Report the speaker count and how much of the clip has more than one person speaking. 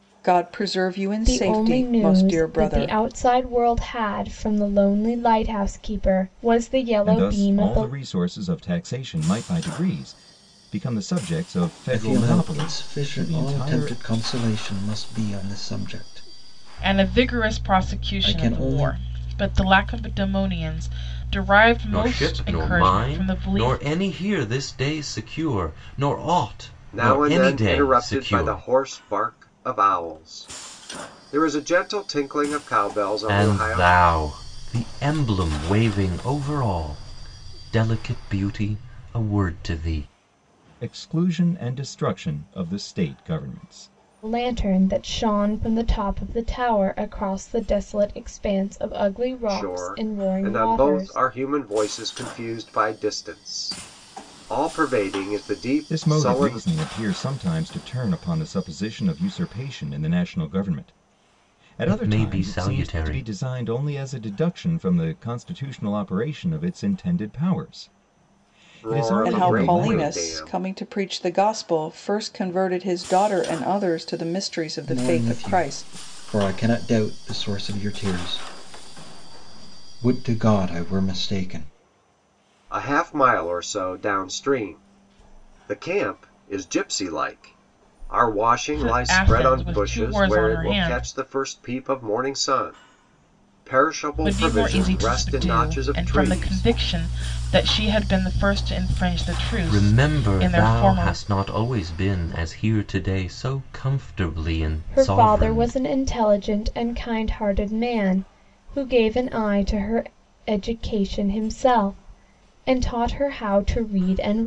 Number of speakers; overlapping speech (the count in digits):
7, about 22%